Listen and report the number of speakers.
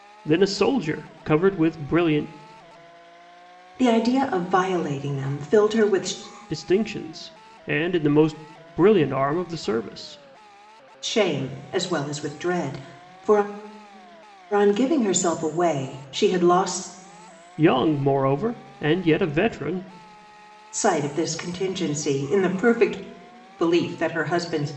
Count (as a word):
two